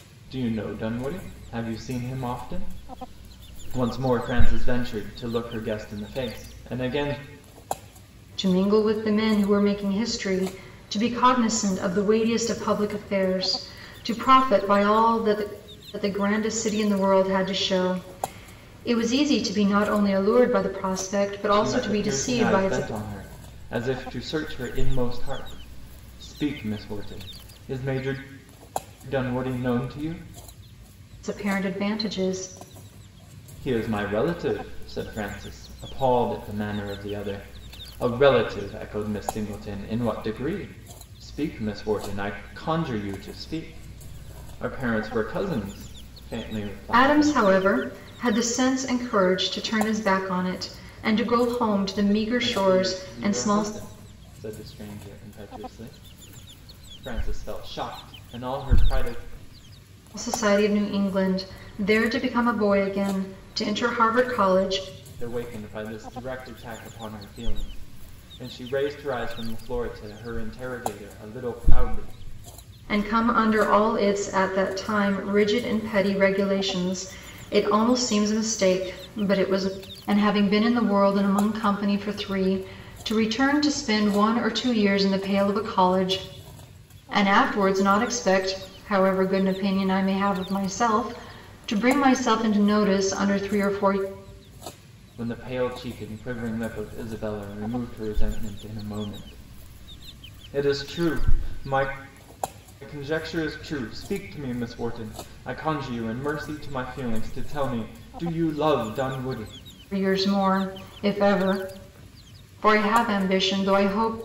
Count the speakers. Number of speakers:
2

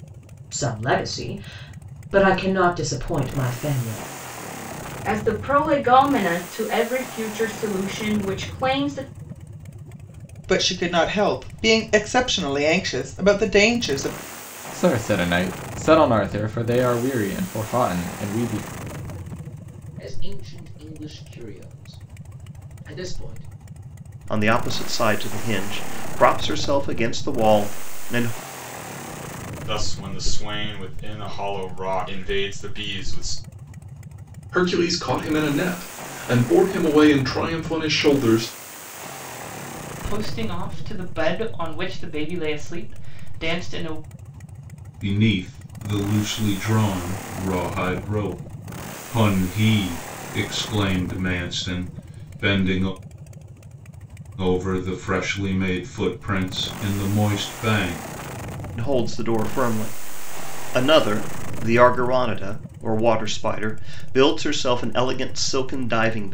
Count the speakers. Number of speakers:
10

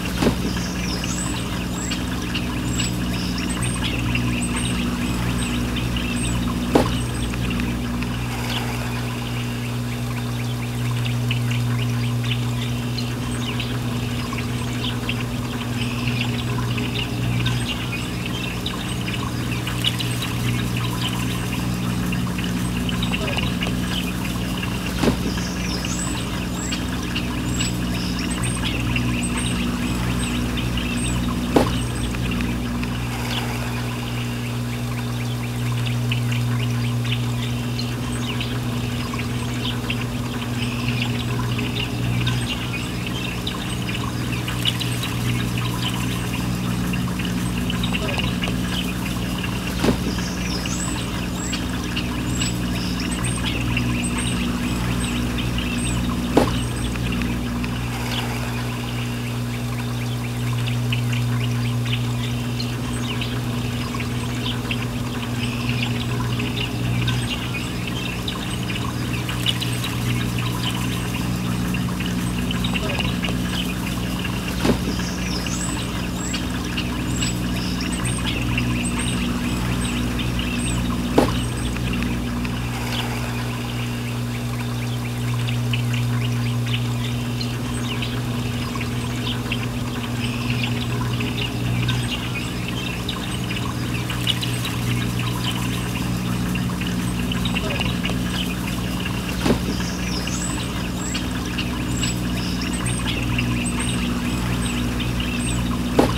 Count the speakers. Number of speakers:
0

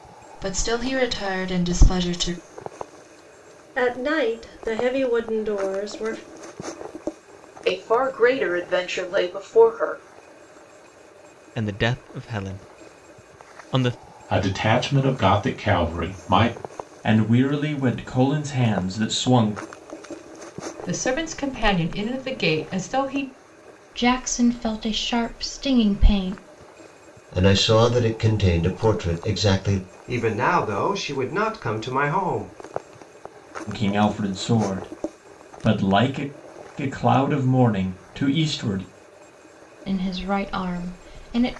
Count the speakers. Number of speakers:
10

